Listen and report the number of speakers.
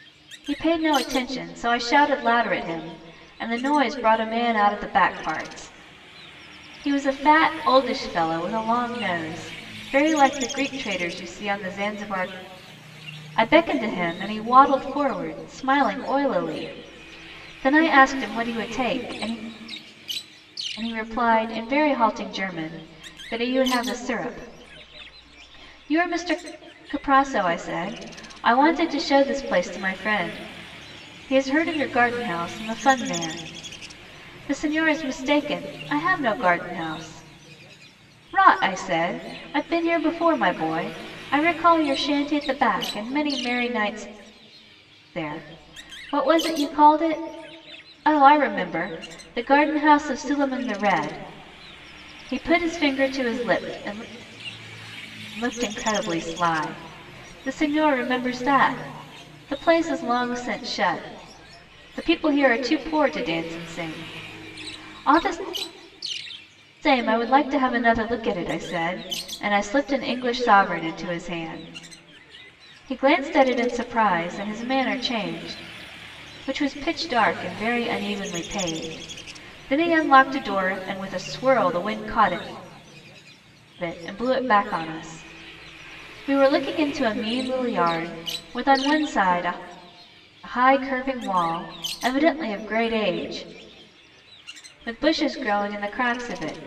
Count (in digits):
1